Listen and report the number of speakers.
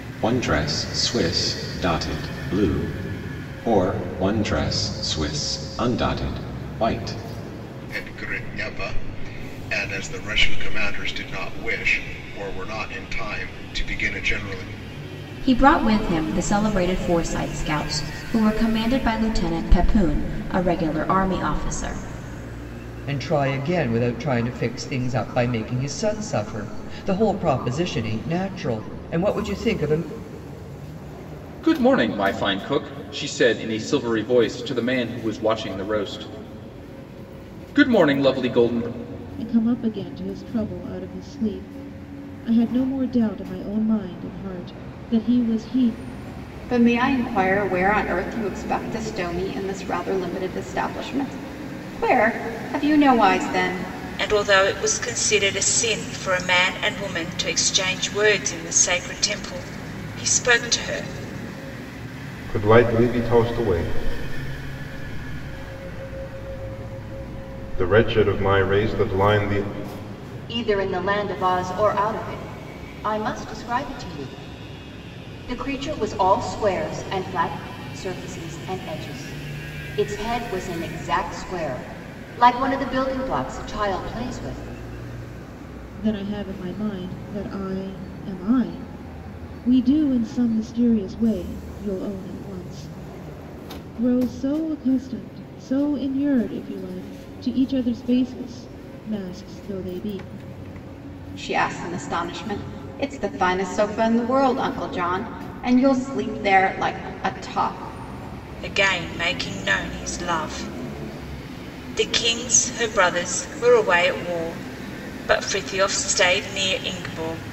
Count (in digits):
10